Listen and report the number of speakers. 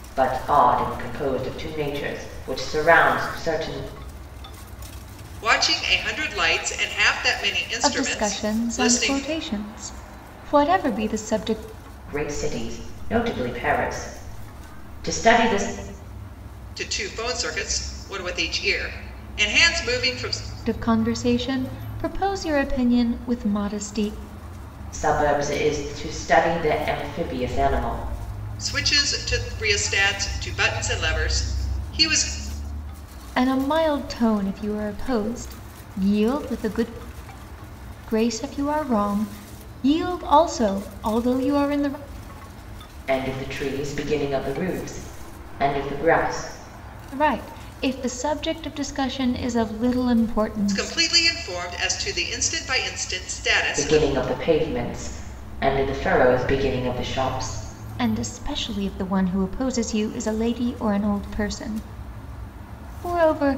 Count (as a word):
three